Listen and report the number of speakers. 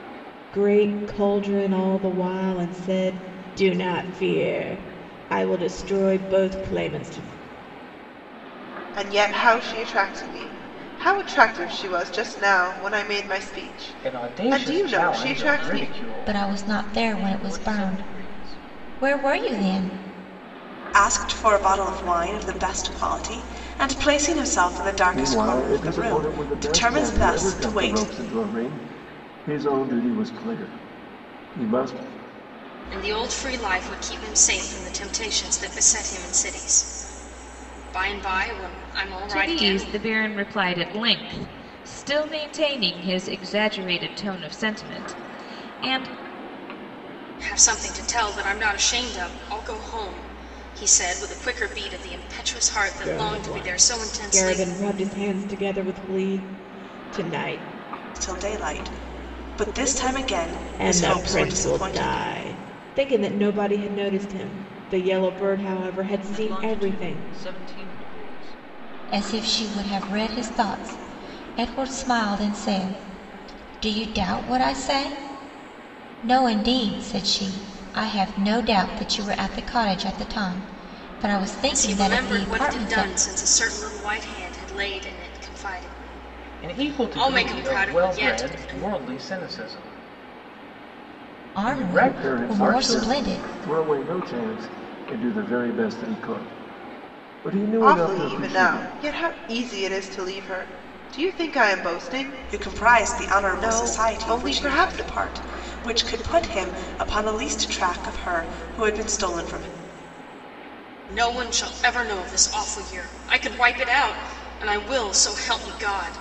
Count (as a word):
nine